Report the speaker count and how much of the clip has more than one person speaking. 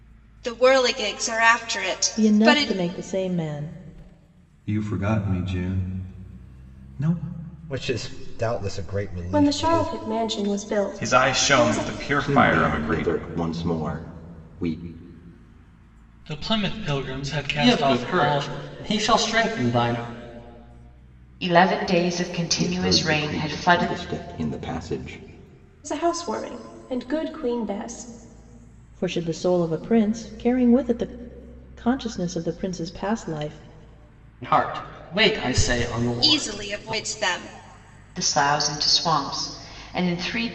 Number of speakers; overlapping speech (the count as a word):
ten, about 16%